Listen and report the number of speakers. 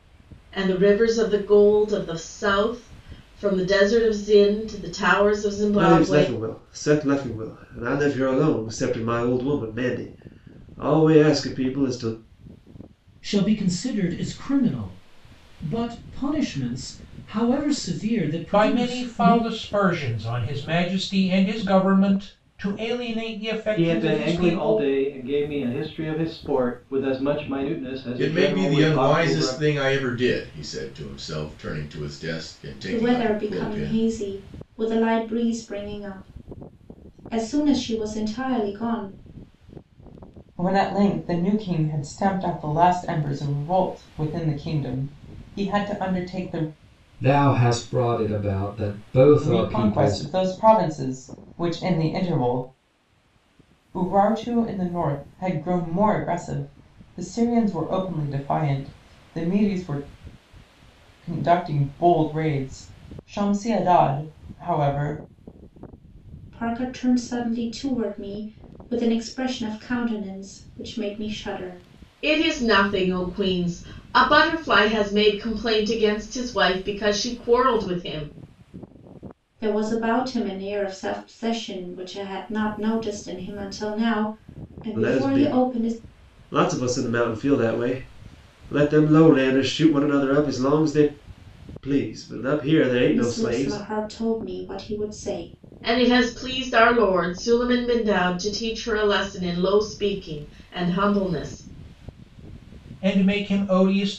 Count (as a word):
nine